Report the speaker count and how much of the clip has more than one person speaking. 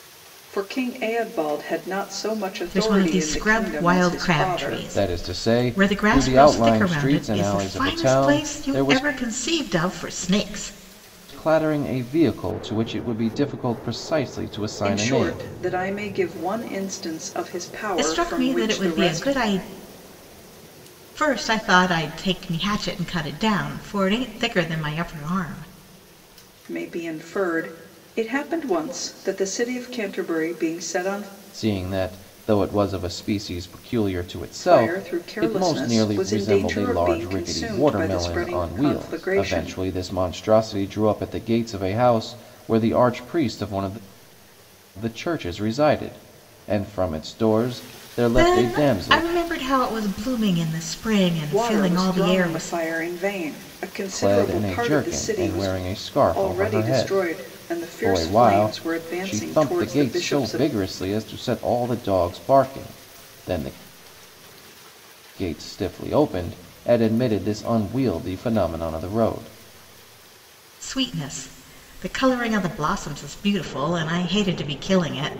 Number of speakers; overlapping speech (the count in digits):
3, about 29%